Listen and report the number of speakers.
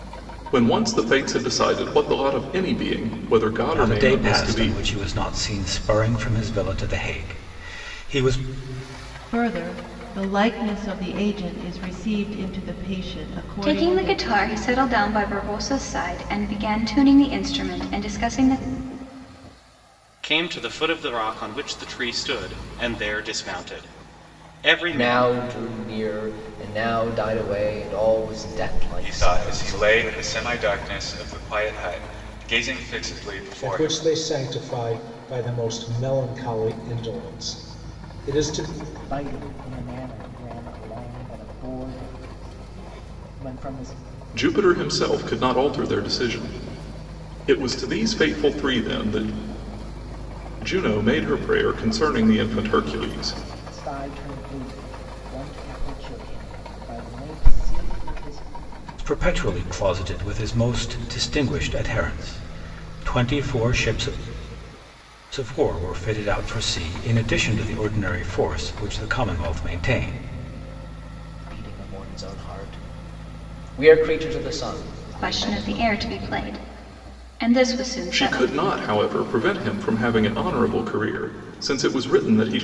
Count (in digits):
9